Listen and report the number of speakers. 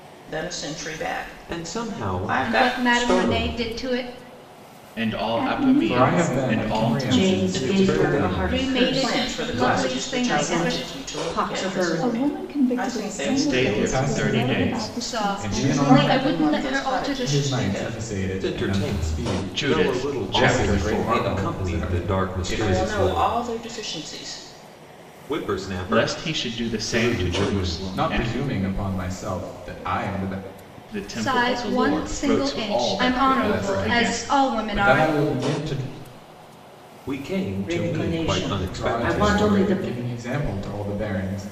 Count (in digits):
7